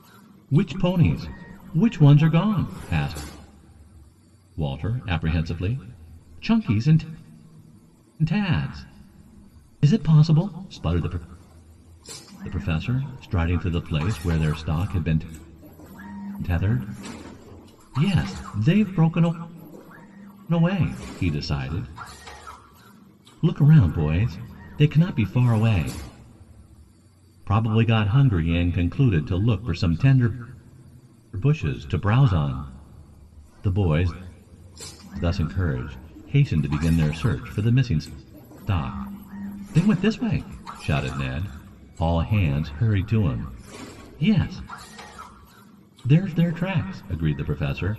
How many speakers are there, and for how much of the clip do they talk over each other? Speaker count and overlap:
1, no overlap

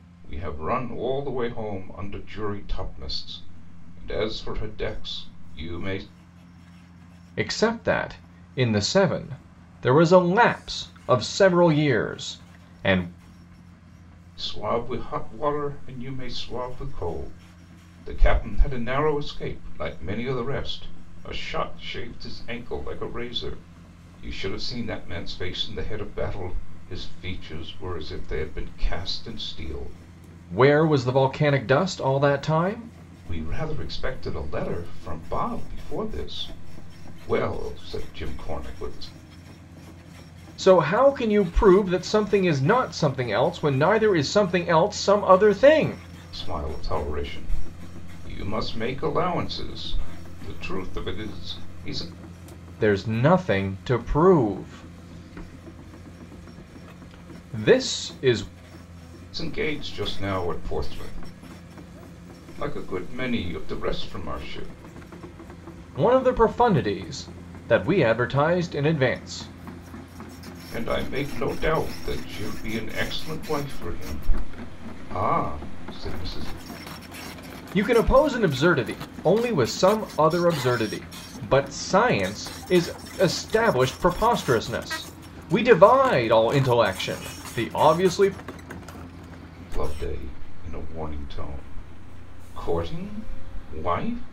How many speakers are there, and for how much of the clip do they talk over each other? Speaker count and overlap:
2, no overlap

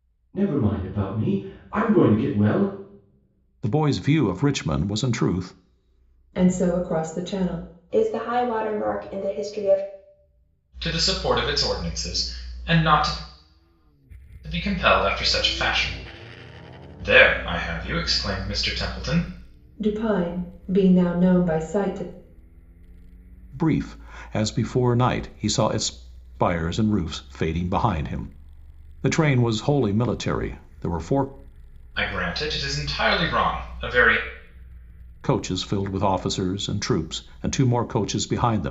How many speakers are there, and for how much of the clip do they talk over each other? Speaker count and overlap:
5, no overlap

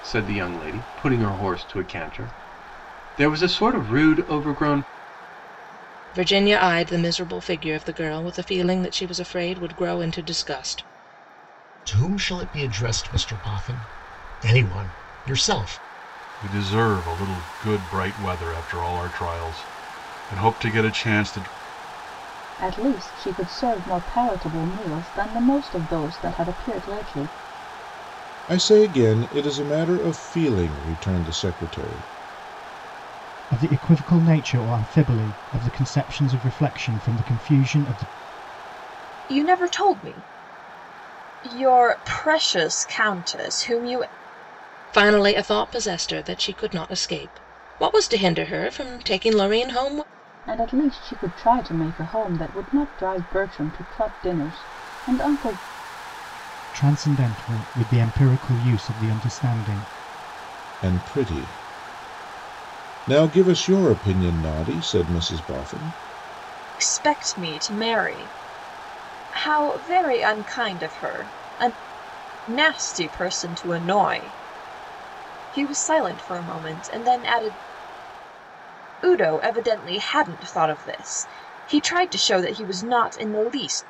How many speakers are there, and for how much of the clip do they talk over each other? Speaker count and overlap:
8, no overlap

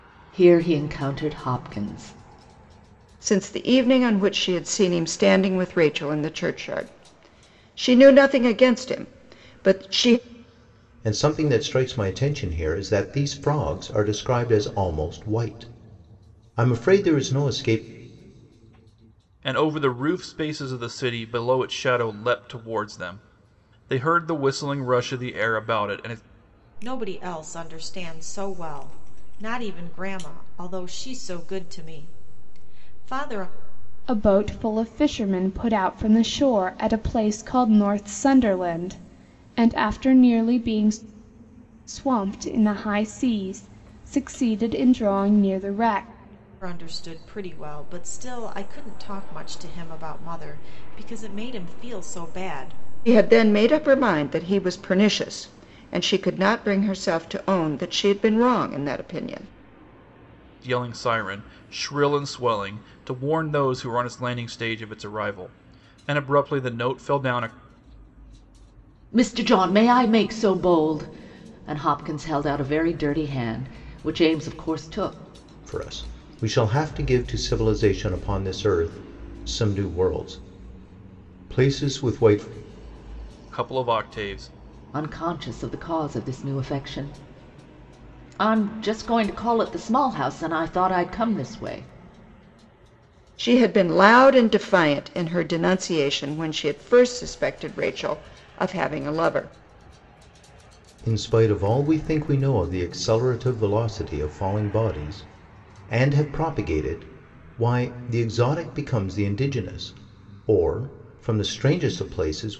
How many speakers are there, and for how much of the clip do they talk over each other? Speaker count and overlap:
6, no overlap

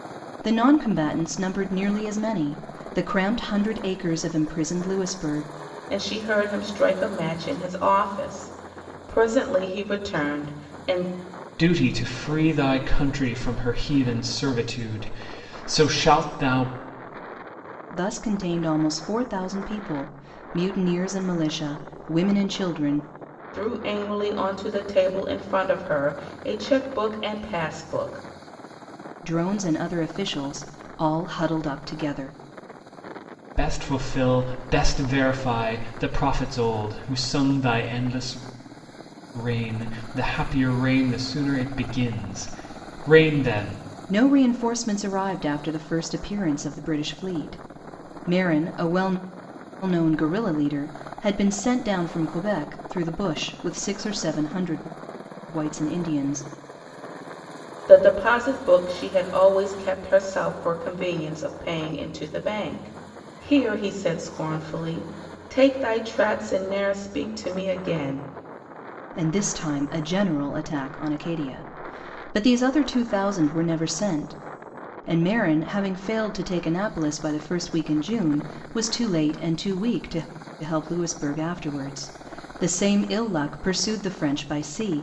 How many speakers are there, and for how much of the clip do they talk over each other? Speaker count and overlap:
3, no overlap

